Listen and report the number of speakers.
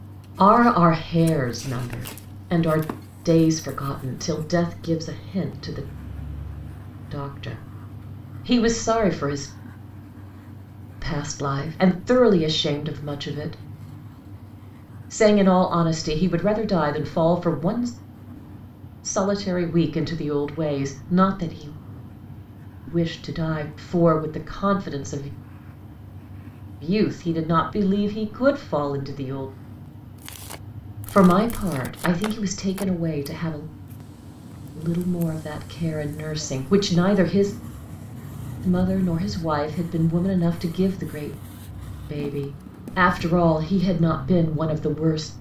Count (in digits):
1